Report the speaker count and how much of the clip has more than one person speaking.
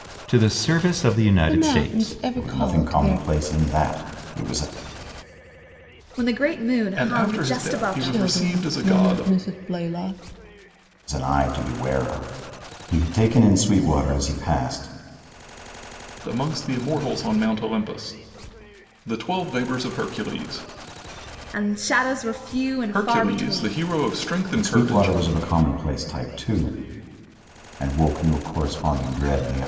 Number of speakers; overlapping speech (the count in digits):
5, about 20%